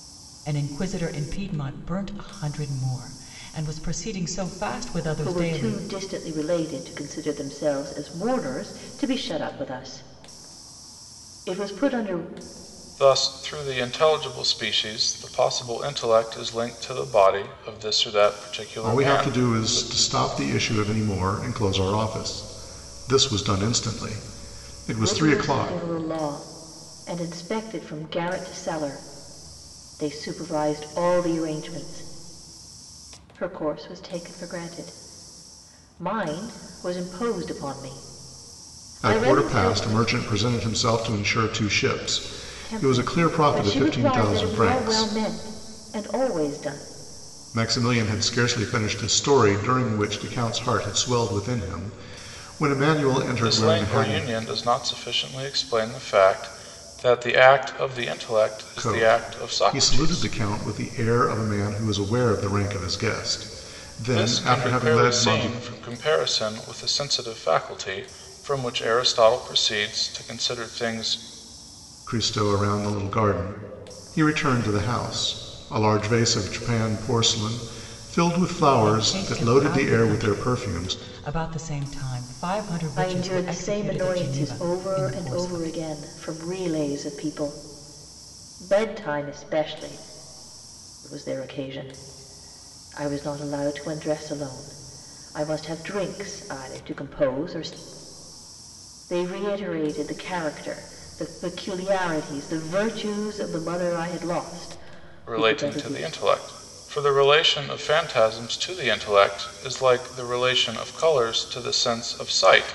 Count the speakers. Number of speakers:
4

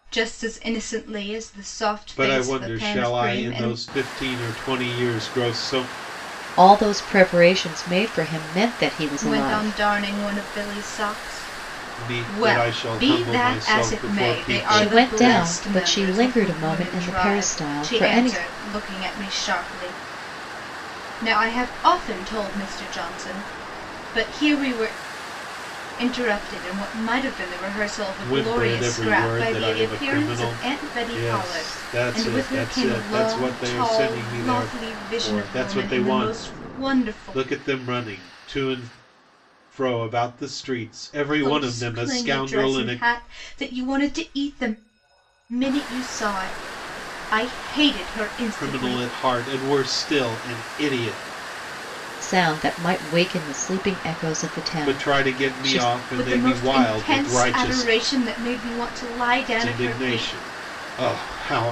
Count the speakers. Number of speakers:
3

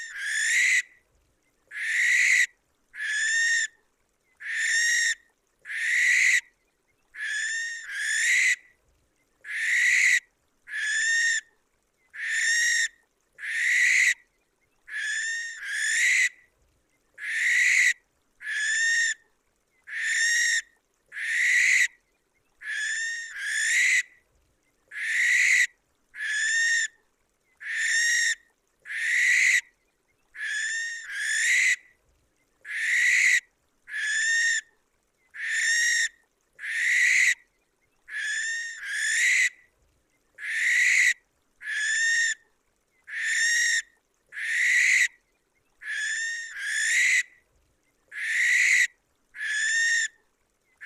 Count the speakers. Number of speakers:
0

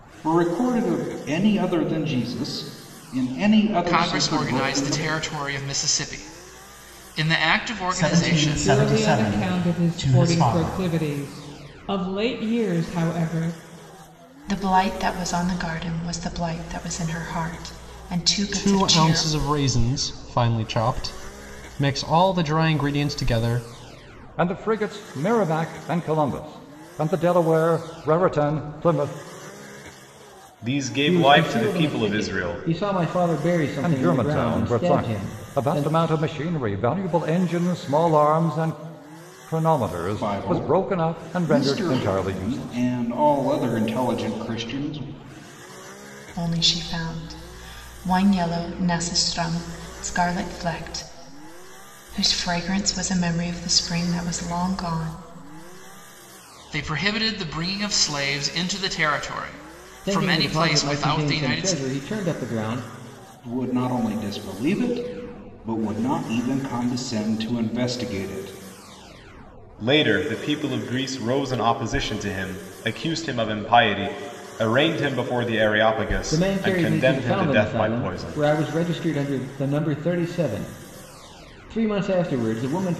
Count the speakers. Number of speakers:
9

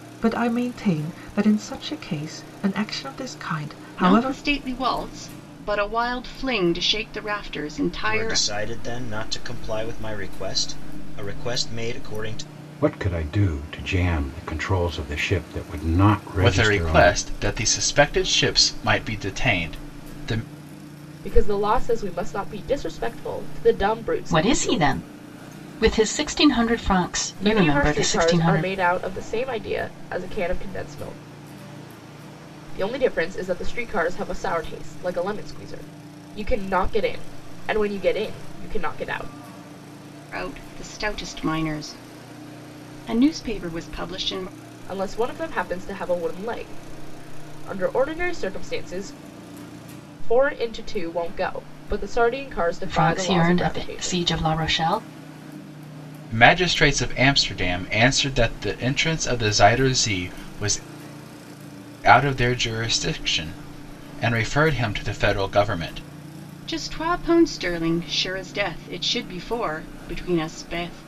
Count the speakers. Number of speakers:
7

